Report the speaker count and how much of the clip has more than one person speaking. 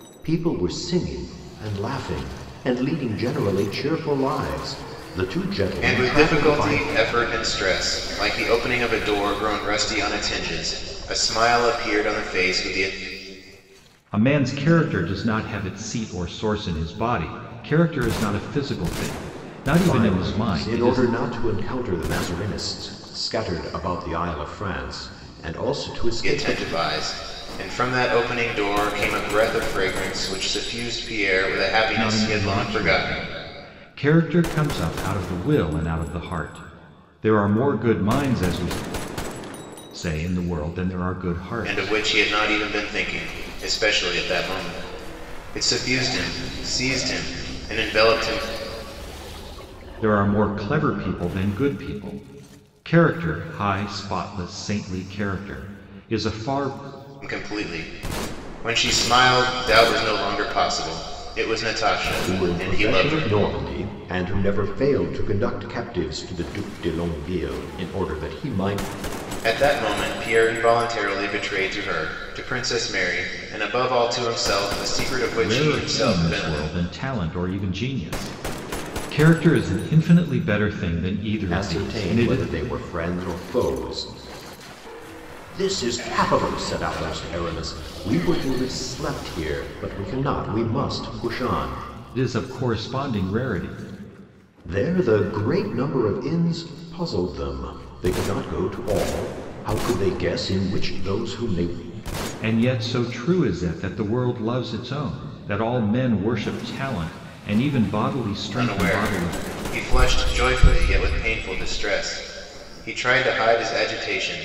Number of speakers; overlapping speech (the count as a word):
three, about 7%